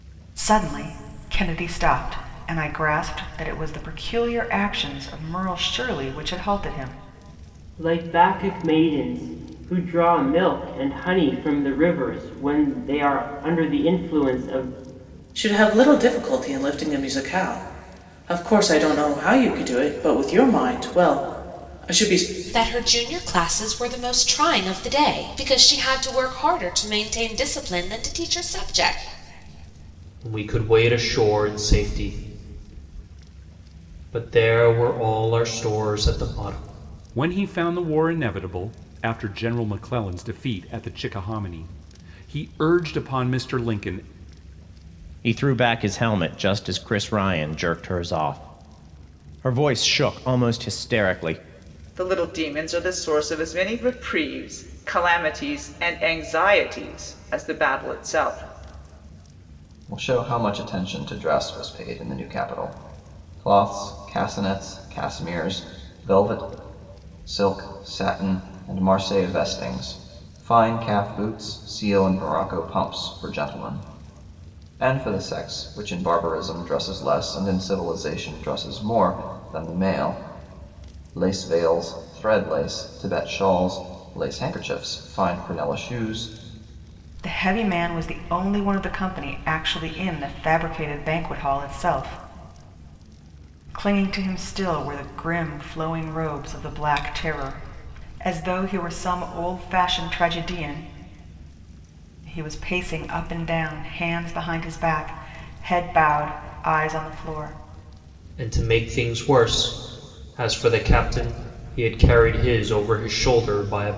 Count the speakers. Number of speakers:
nine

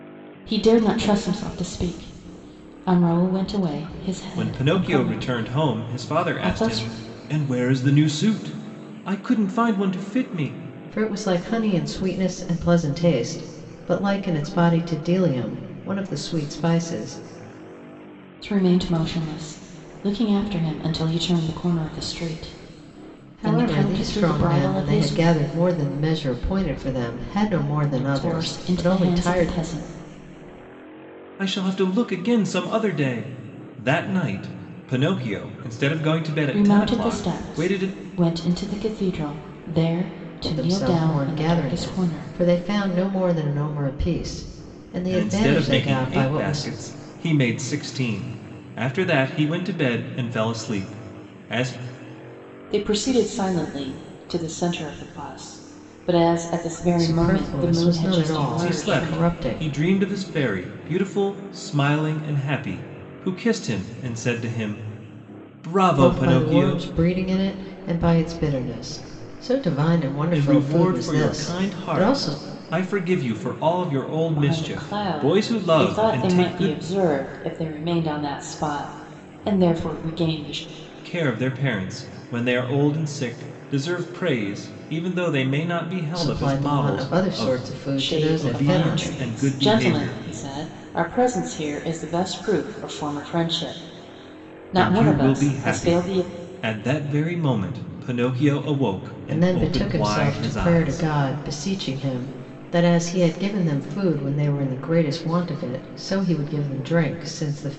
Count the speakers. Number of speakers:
three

